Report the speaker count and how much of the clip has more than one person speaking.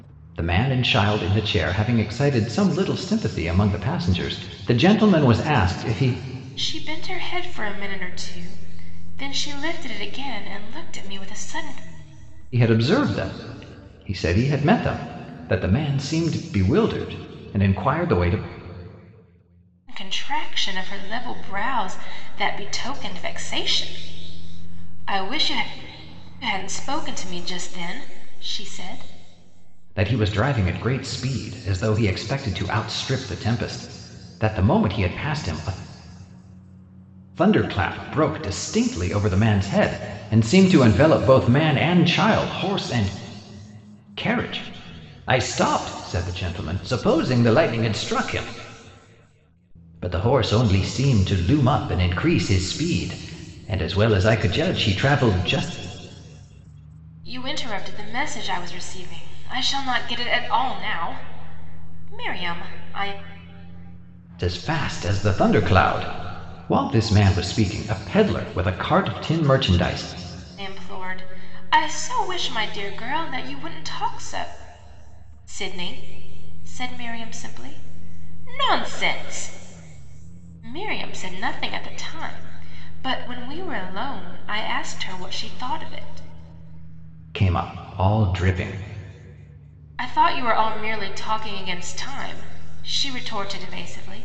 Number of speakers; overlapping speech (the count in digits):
2, no overlap